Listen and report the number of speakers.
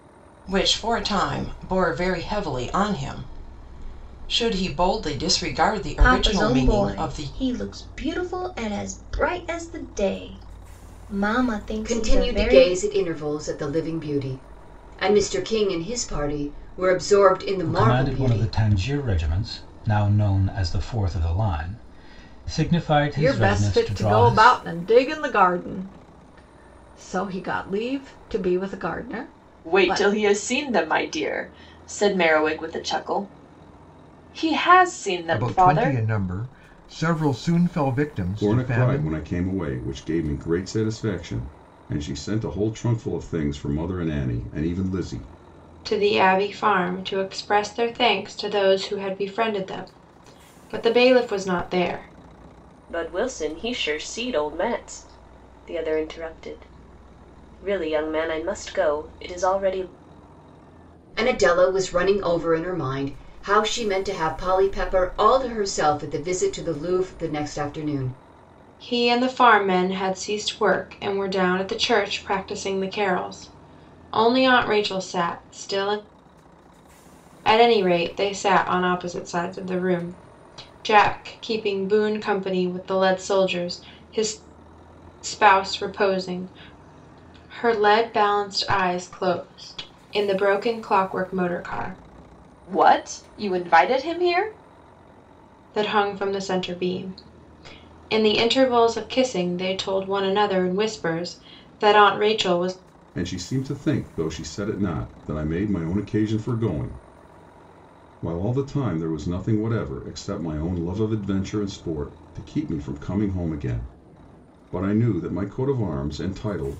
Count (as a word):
ten